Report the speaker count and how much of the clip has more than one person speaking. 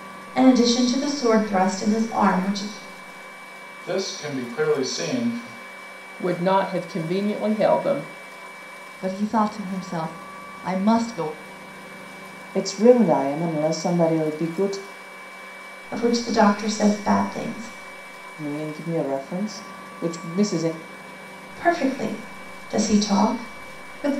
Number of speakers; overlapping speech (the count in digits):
5, no overlap